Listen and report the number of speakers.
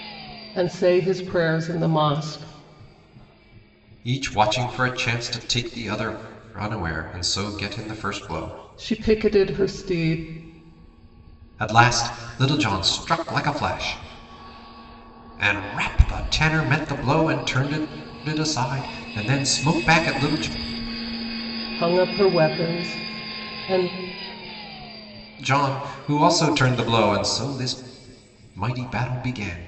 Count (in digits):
2